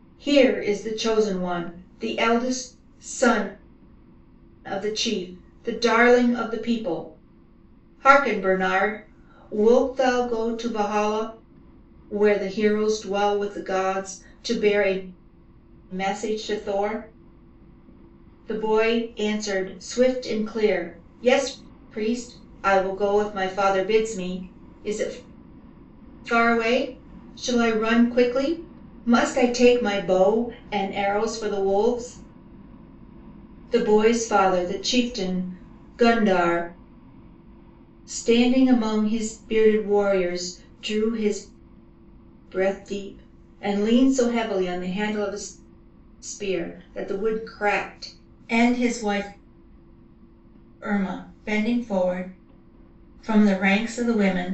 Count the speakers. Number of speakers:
1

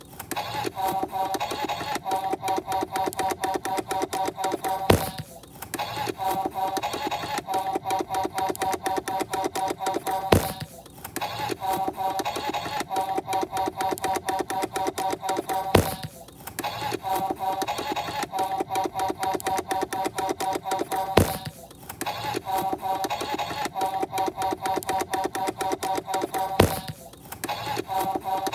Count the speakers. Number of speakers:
0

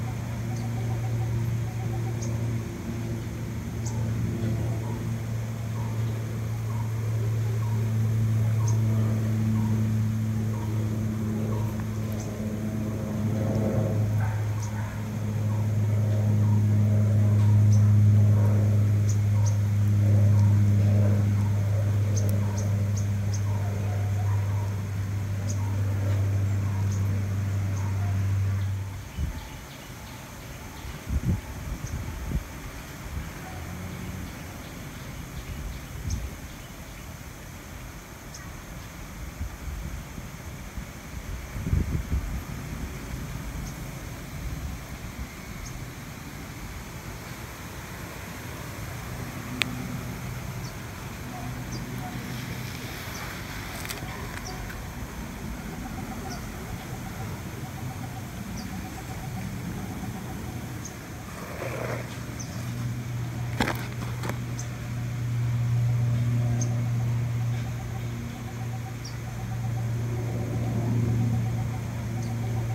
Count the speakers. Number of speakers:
0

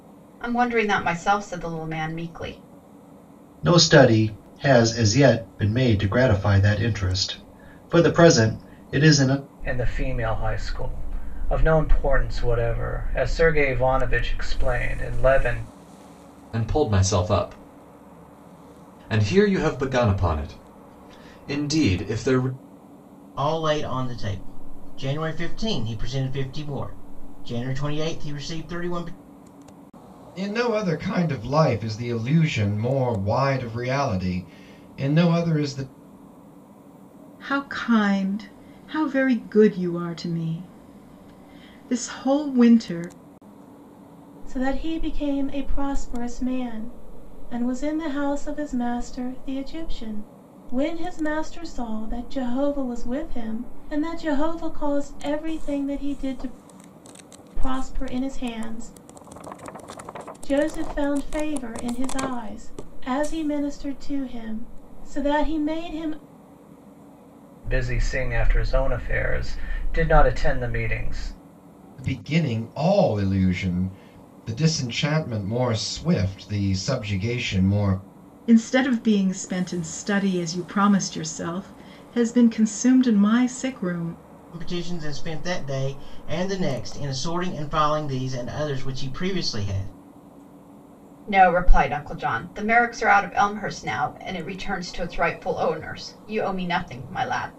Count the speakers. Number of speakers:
8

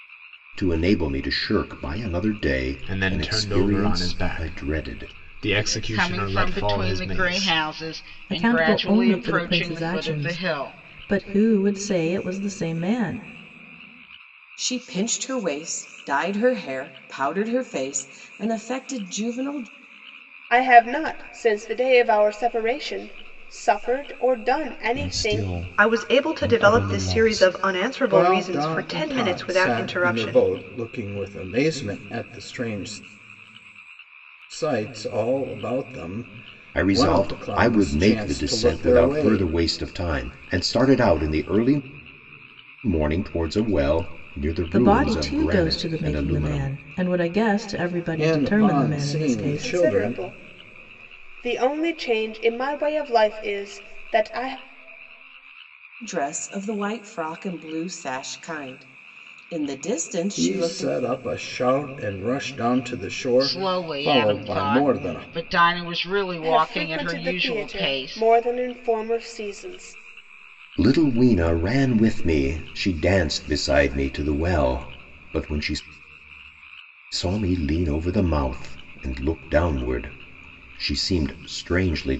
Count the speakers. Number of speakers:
9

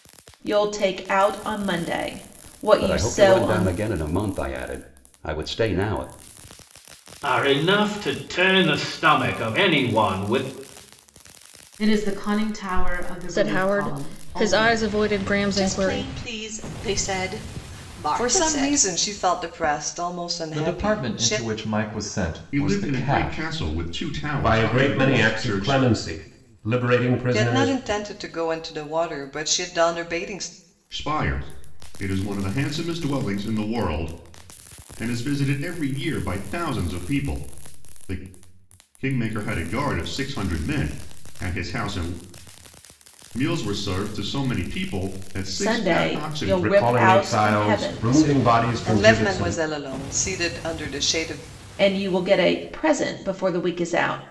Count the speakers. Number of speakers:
10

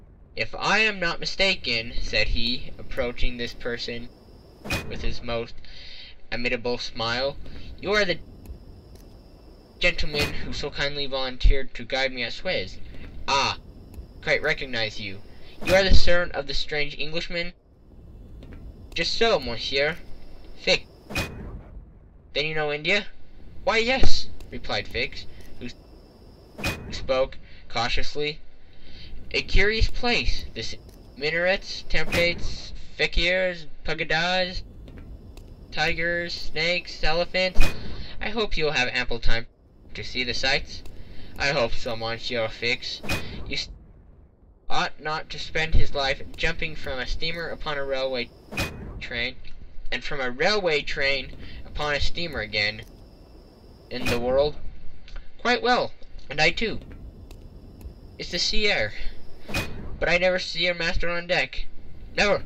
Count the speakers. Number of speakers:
1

